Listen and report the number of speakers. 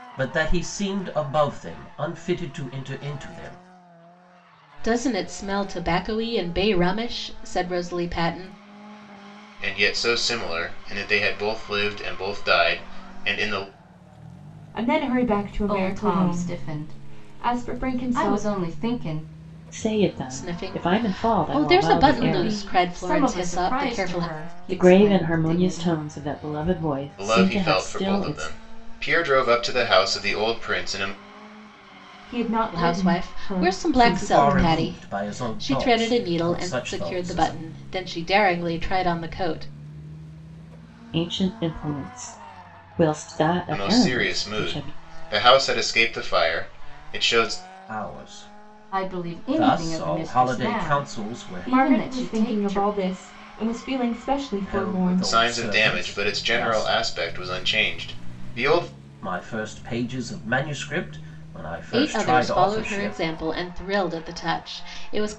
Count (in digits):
6